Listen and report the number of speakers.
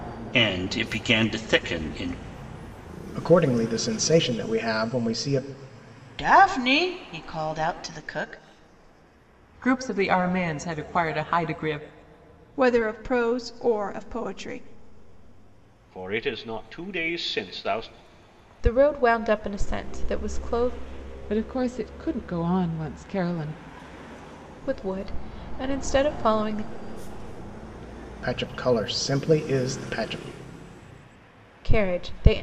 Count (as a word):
eight